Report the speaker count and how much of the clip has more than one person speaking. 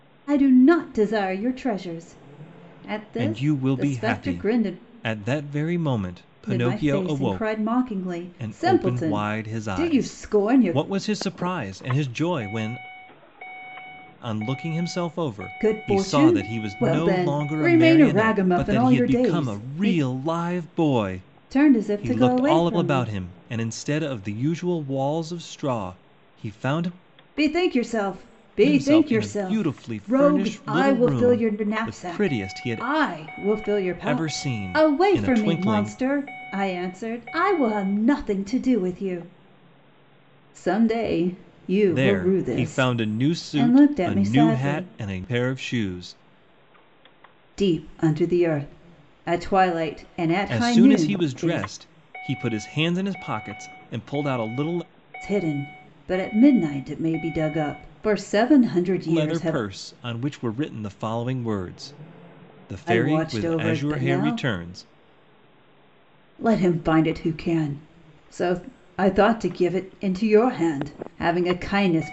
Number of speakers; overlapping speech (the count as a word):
two, about 33%